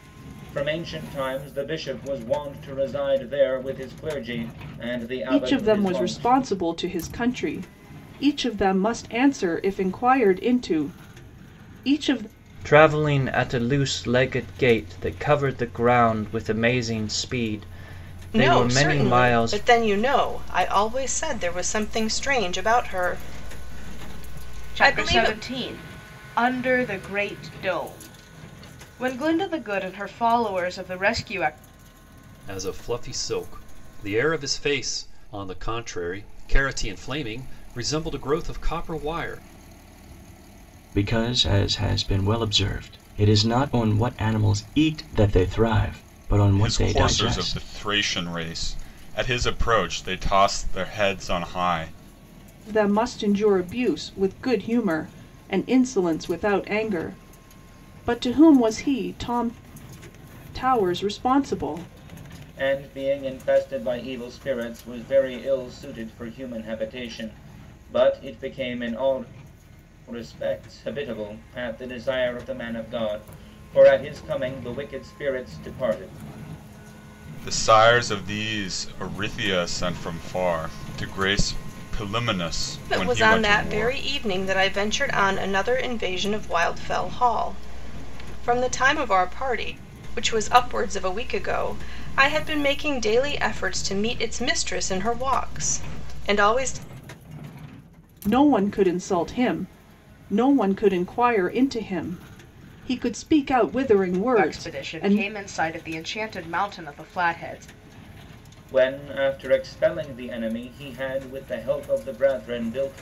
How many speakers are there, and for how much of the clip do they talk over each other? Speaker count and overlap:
8, about 5%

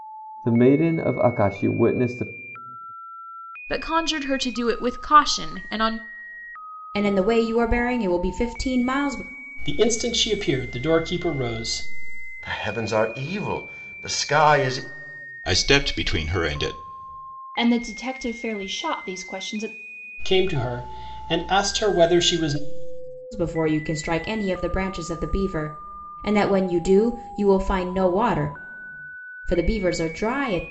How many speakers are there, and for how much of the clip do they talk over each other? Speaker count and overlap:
7, no overlap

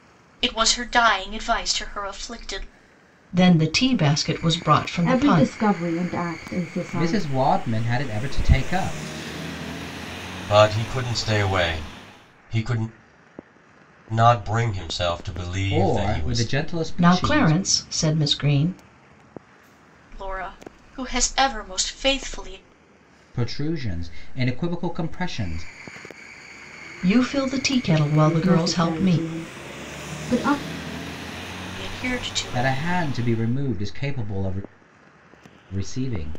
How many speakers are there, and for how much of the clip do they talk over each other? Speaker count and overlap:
5, about 10%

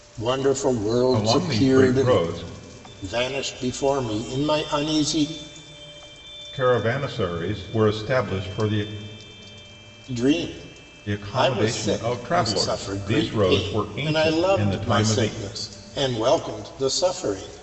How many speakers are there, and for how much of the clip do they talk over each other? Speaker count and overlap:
2, about 30%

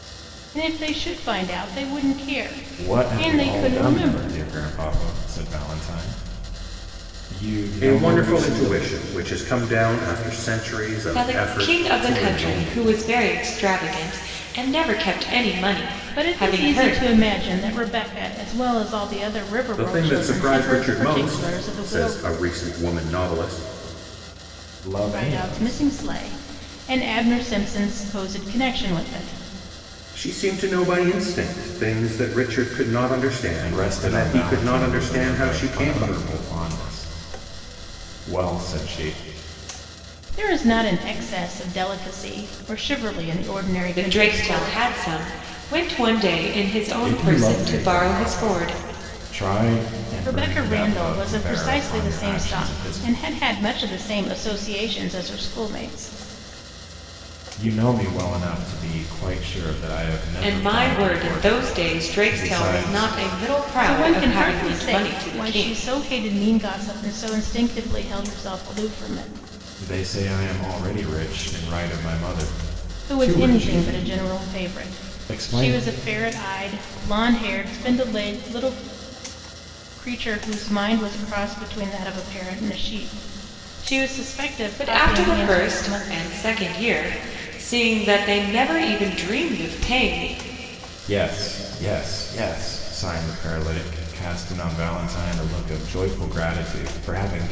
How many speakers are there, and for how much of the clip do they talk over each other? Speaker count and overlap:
4, about 26%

